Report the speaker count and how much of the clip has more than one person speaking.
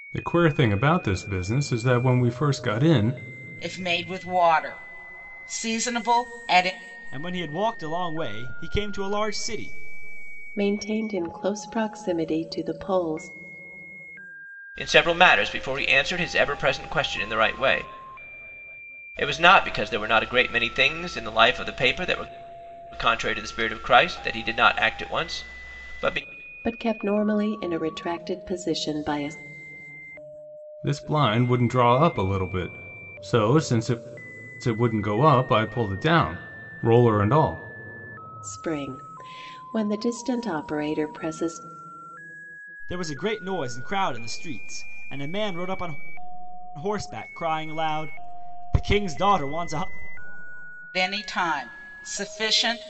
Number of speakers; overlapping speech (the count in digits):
5, no overlap